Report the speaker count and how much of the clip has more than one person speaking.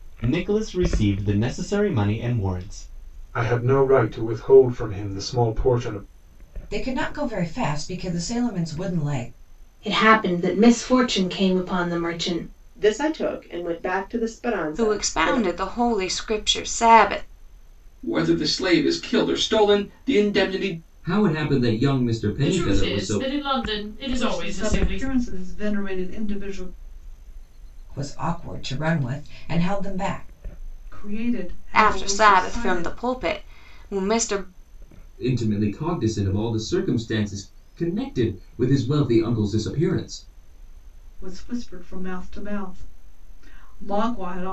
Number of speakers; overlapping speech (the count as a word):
ten, about 9%